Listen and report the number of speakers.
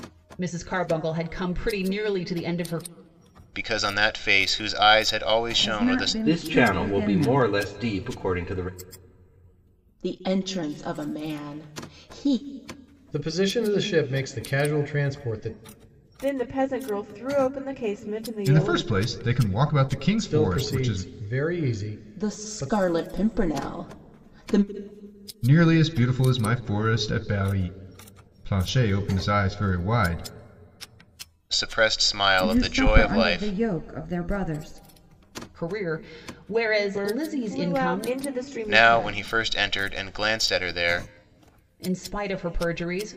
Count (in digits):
8